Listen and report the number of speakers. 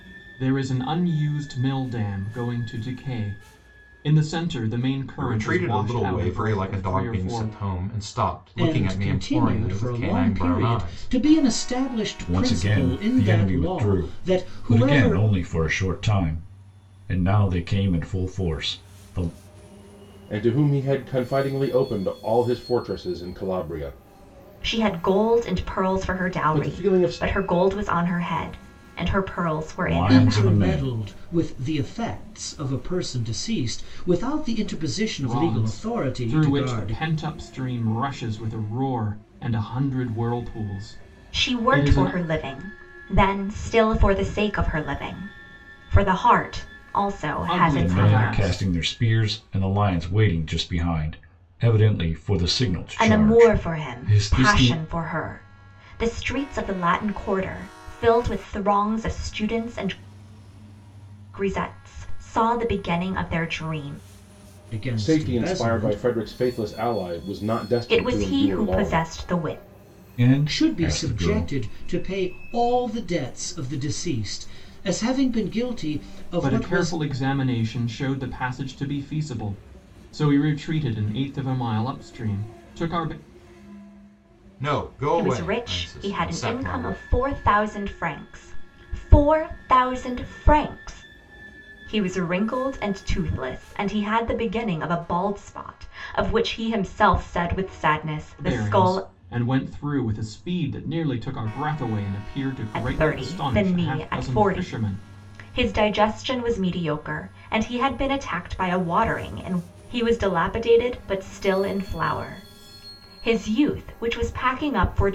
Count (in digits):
6